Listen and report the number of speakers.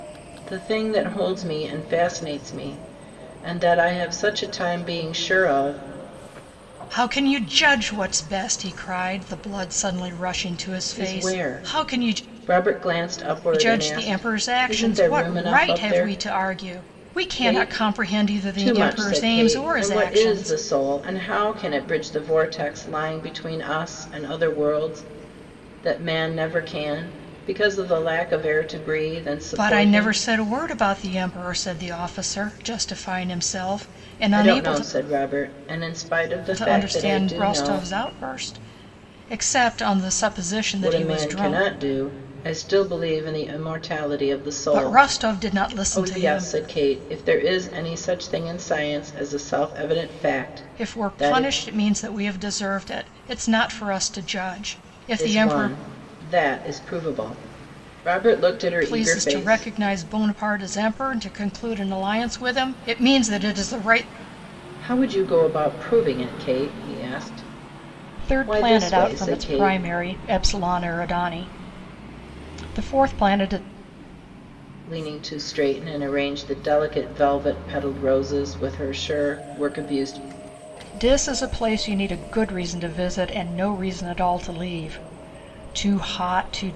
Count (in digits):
2